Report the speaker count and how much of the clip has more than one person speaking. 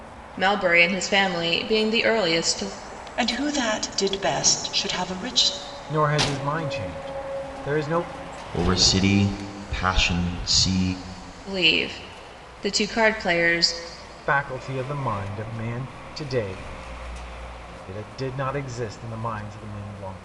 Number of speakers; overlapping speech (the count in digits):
4, no overlap